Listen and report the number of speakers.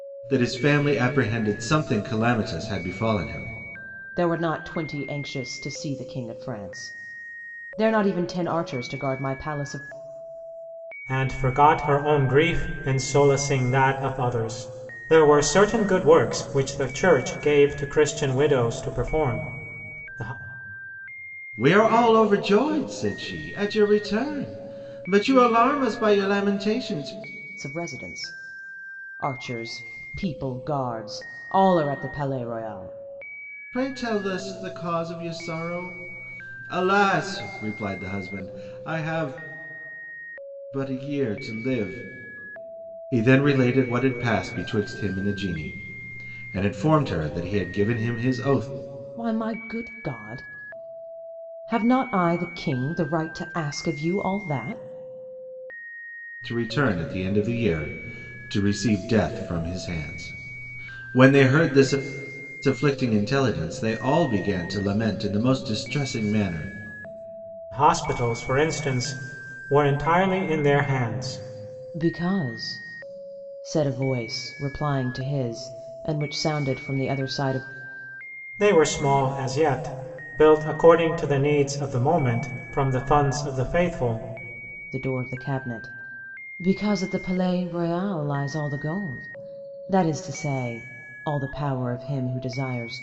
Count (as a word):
three